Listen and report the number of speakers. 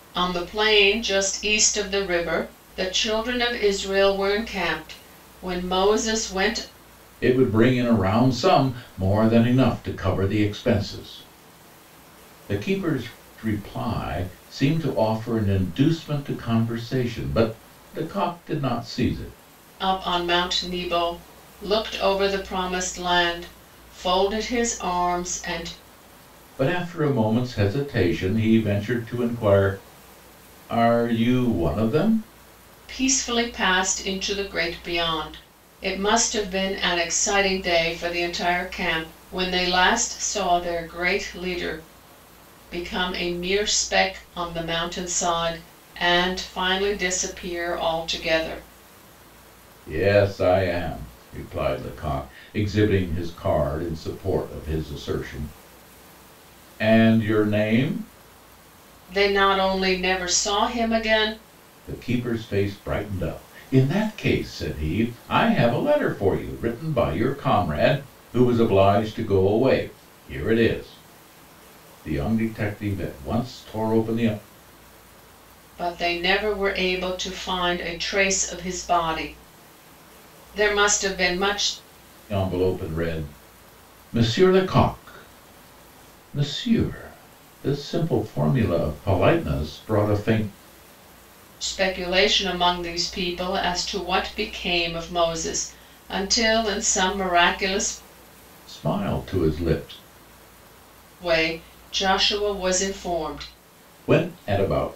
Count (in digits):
2